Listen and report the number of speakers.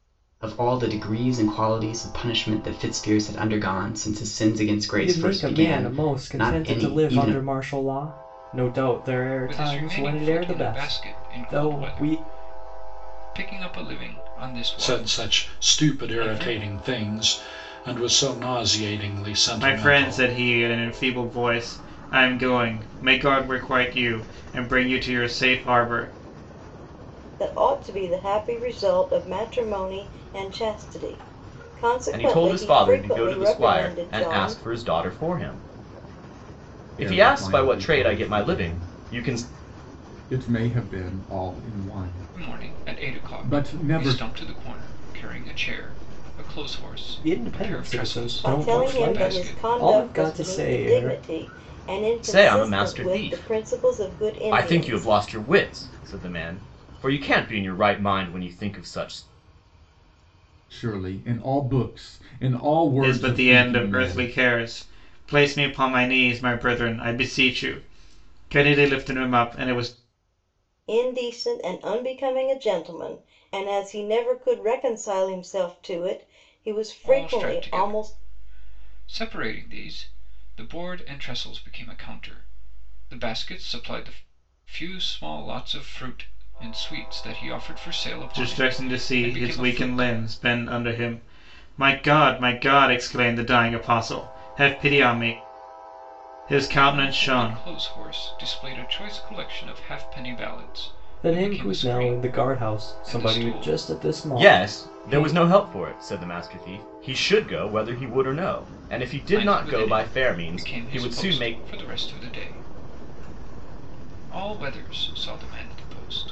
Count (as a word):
eight